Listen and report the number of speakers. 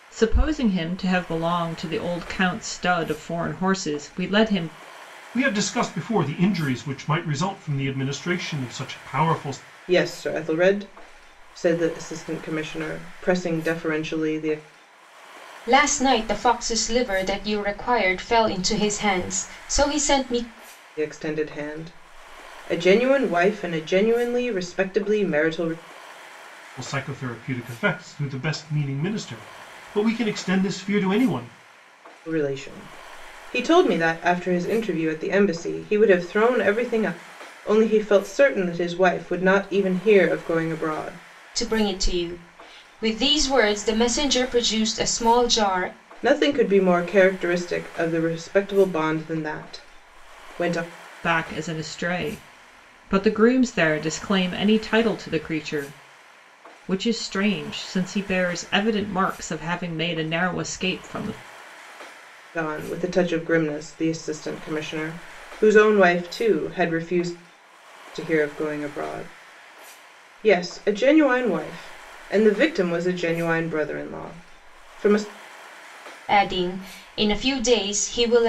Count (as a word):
four